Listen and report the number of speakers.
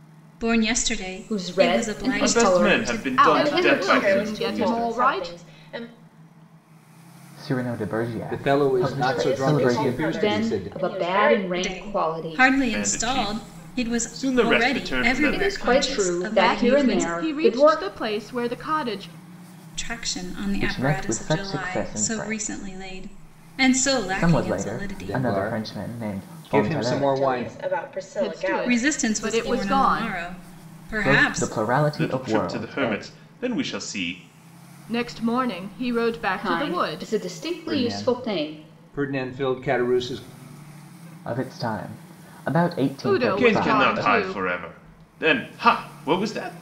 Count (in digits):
7